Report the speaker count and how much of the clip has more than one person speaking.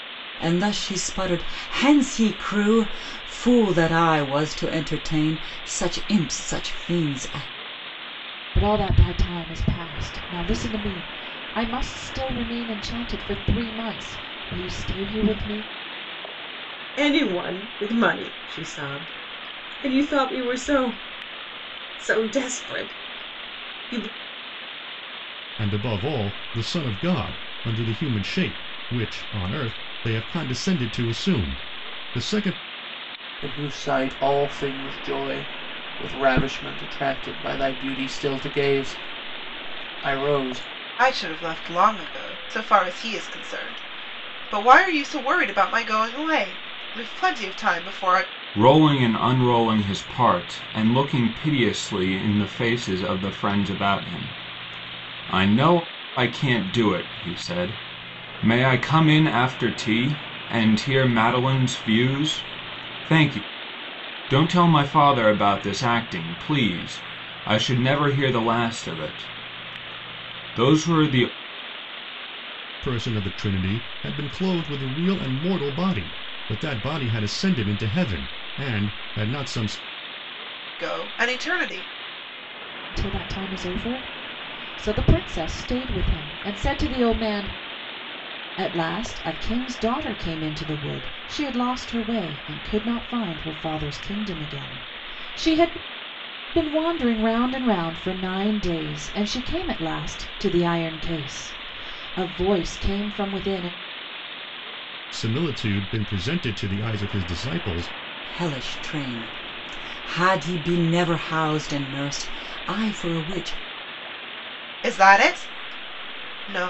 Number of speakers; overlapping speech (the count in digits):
7, no overlap